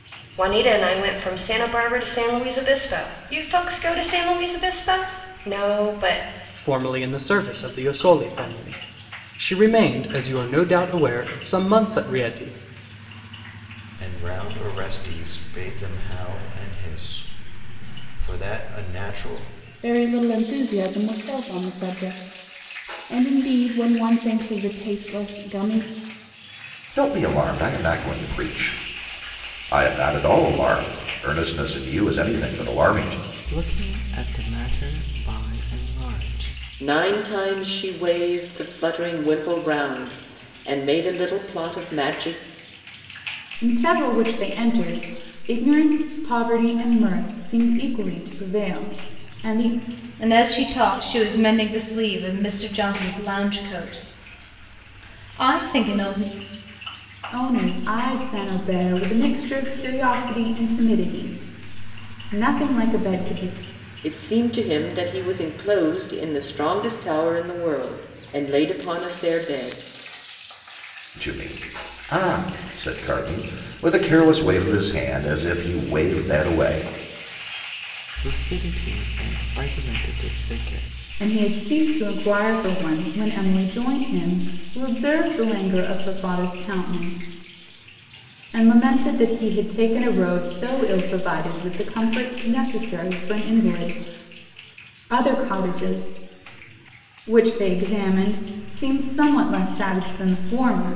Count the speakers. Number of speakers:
nine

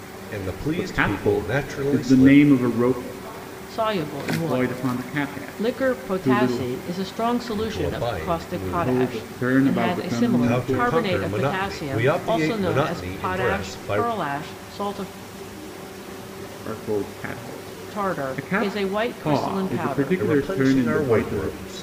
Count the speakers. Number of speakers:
three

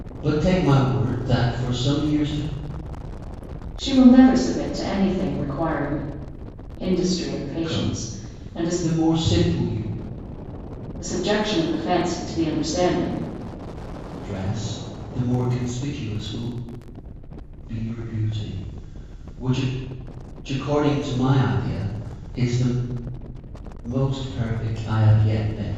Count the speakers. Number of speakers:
two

